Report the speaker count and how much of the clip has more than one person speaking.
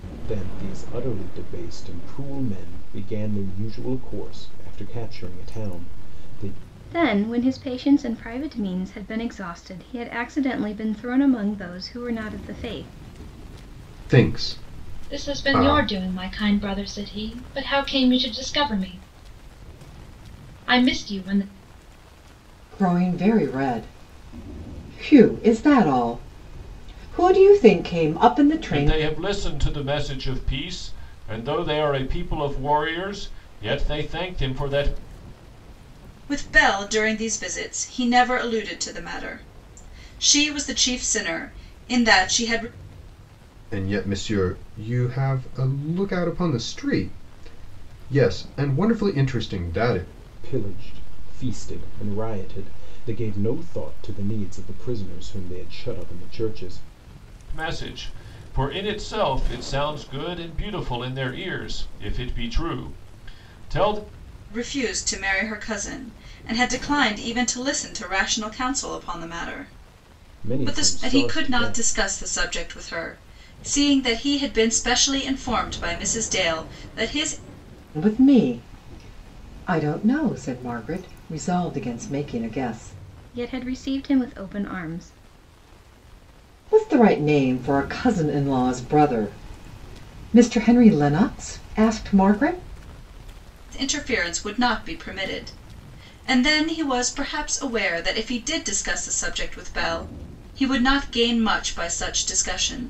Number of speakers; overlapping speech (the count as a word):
seven, about 3%